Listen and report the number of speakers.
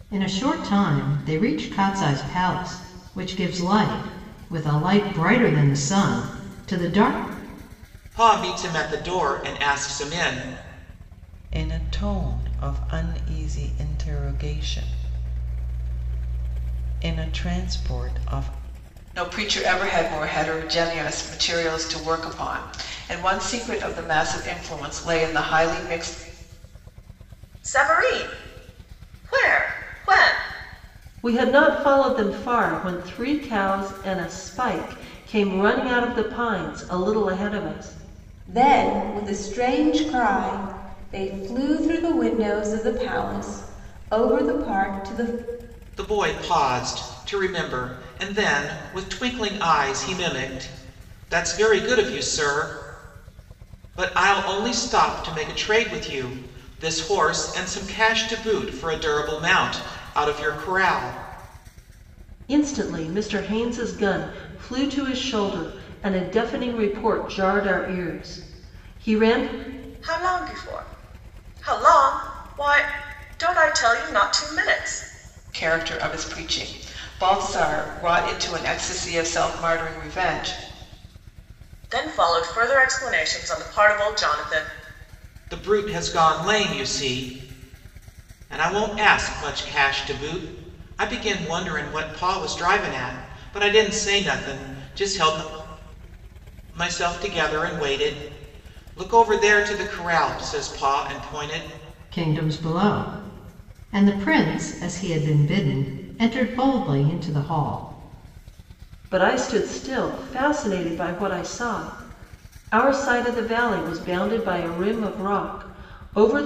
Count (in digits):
7